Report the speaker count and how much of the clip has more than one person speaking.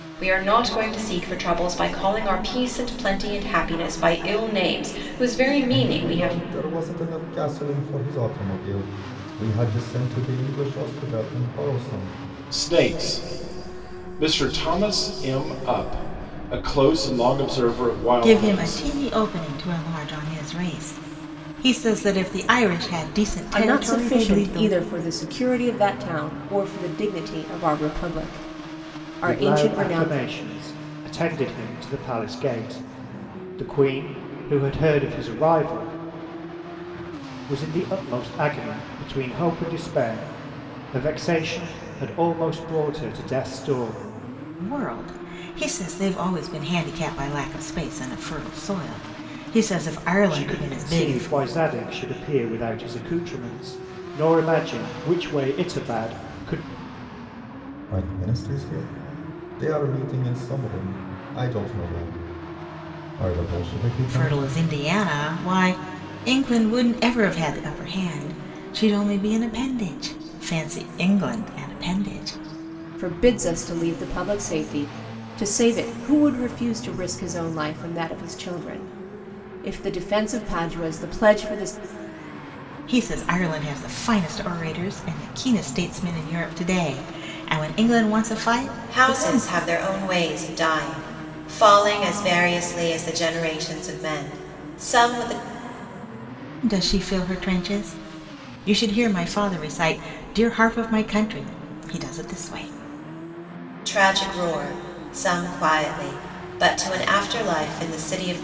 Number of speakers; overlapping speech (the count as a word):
six, about 5%